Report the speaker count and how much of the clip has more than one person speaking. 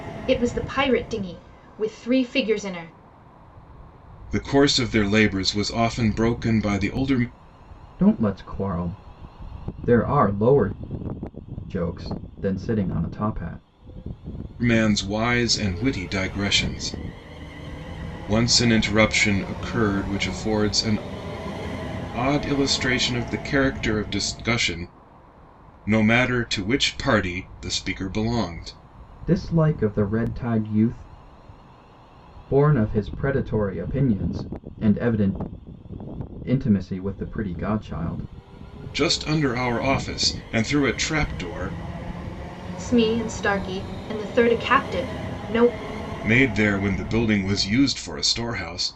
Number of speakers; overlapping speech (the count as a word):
three, no overlap